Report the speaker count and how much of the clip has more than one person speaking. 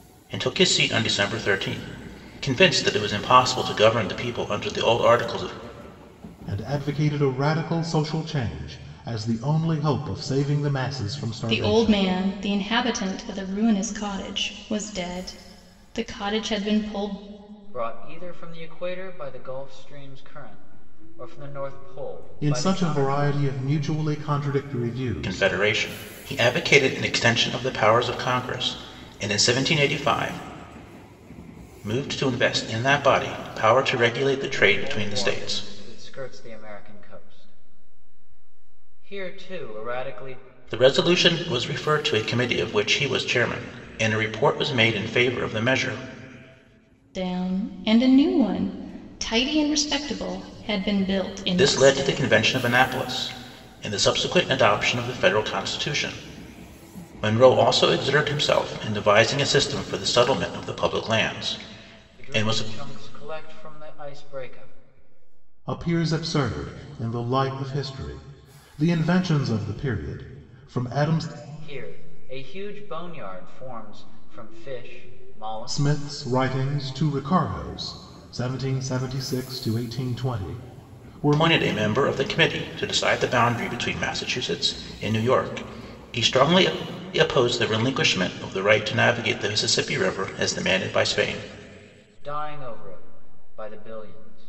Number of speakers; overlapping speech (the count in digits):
4, about 6%